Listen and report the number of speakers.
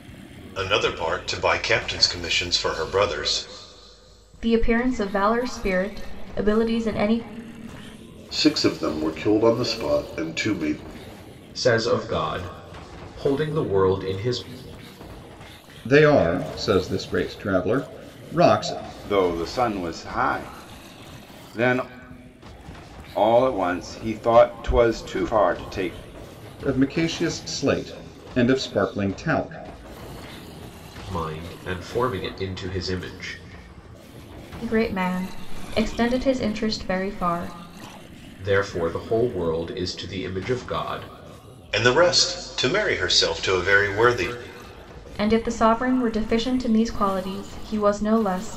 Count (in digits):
6